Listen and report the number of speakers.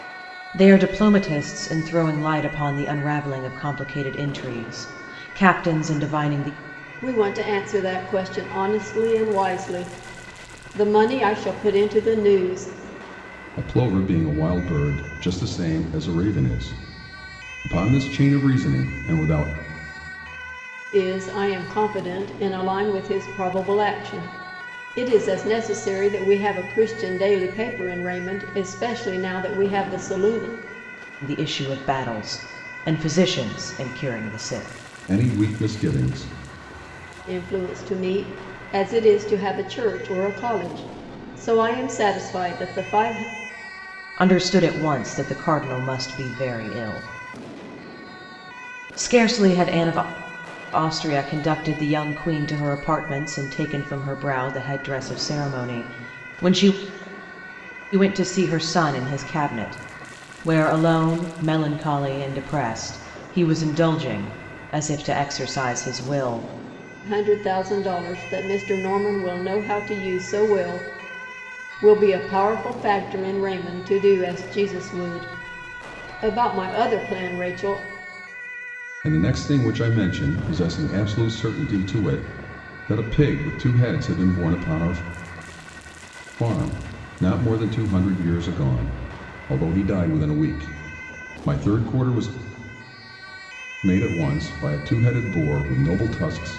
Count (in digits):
3